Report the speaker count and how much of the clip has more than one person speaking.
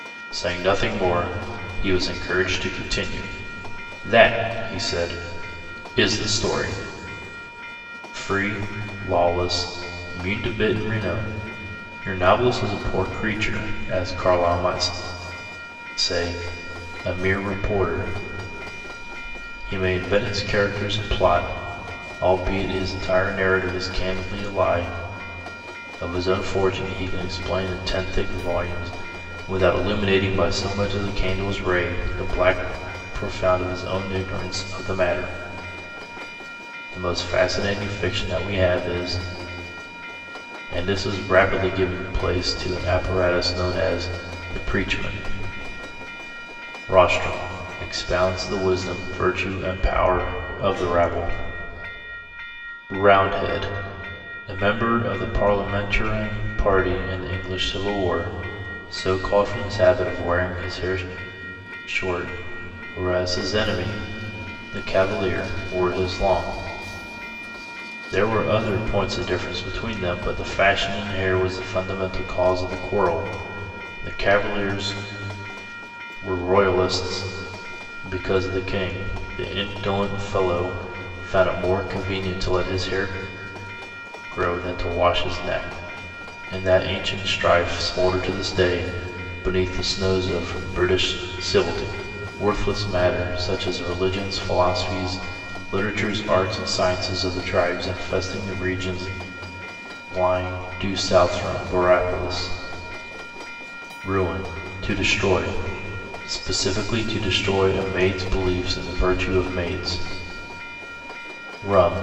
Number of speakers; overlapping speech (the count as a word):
one, no overlap